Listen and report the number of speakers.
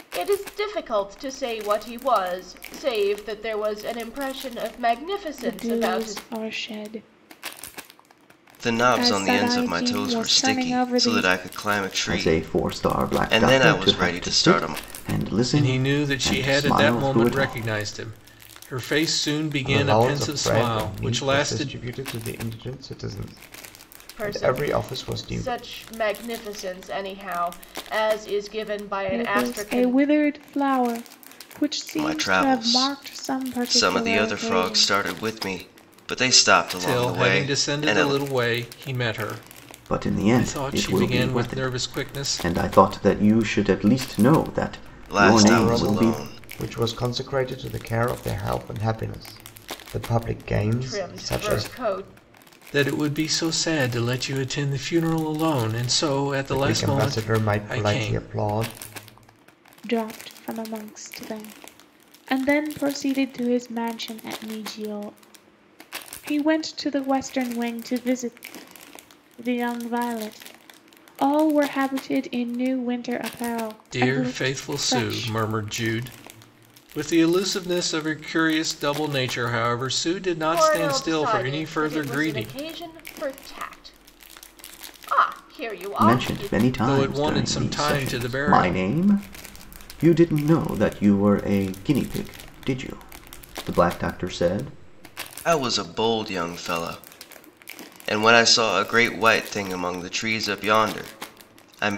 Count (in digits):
6